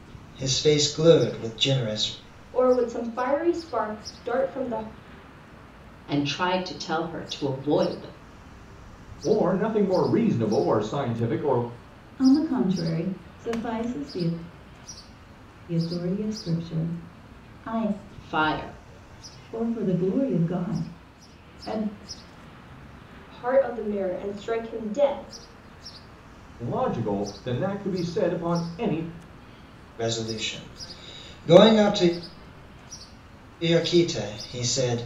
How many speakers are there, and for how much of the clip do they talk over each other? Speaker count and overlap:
5, no overlap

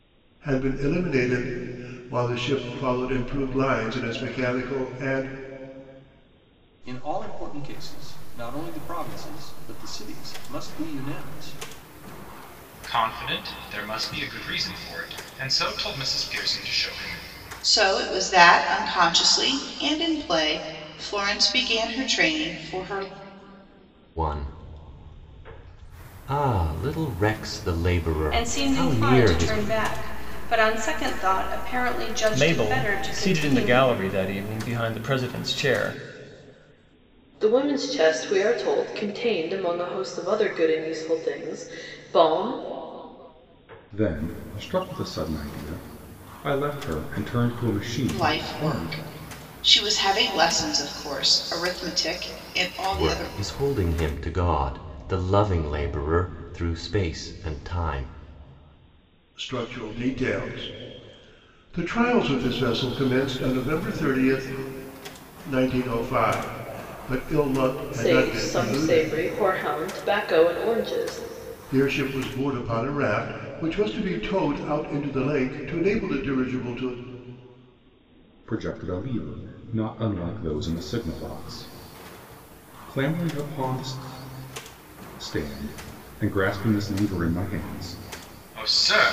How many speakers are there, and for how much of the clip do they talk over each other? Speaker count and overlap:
9, about 6%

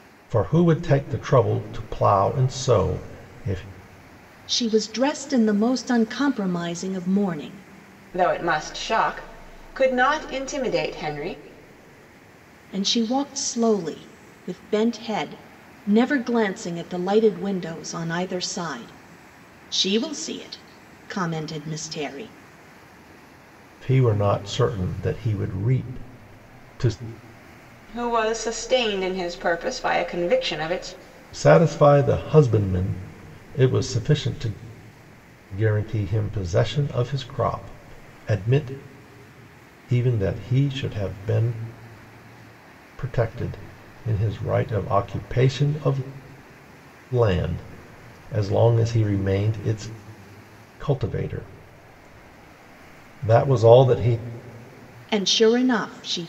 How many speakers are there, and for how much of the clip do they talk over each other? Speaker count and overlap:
3, no overlap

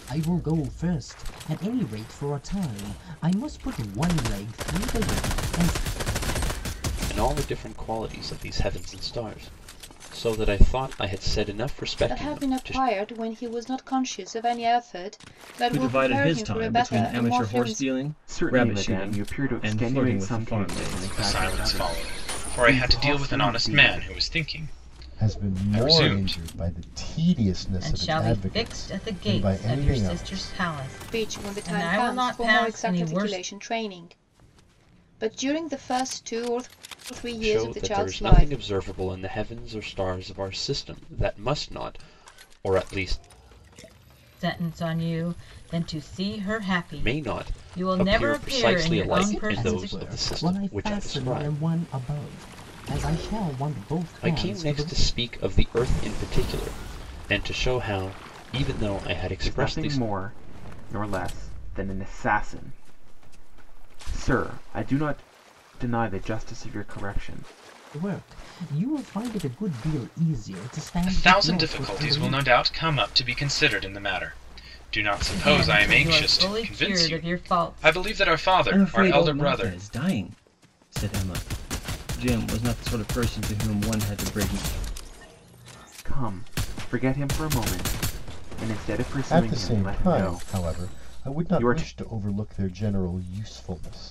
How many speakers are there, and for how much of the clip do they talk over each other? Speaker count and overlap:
8, about 32%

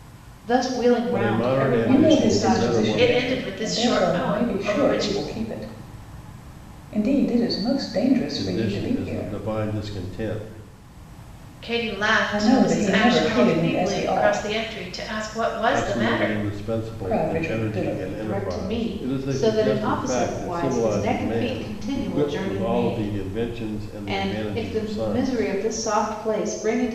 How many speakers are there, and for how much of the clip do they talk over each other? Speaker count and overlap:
4, about 61%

